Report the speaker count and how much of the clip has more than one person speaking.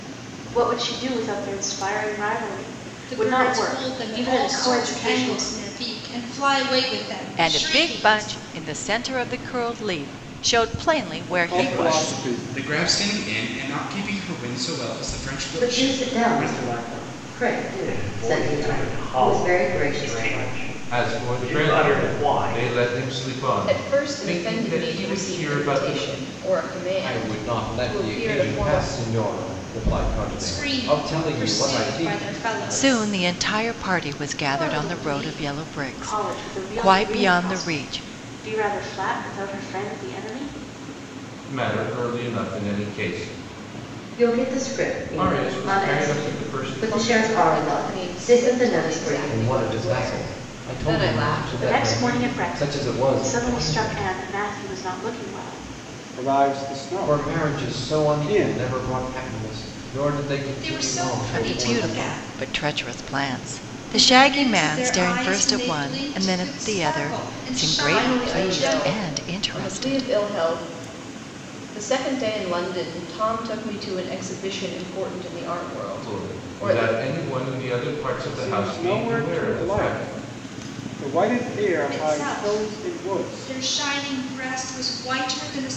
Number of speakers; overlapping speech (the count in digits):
10, about 53%